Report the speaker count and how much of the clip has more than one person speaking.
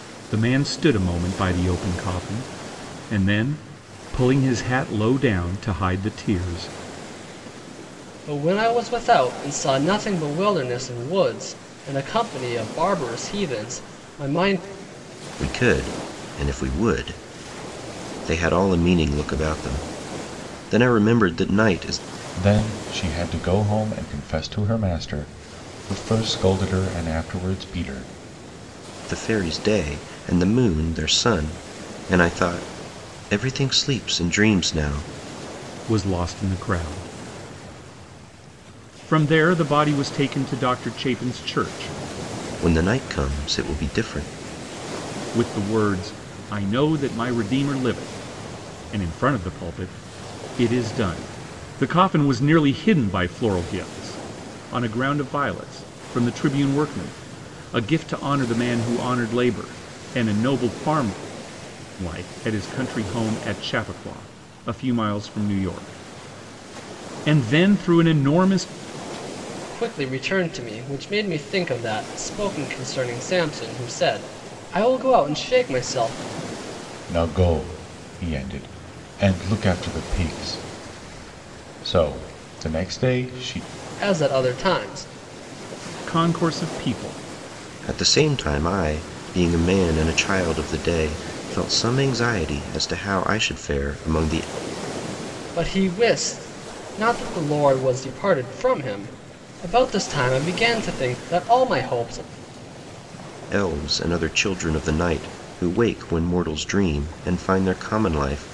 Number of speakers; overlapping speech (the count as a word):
four, no overlap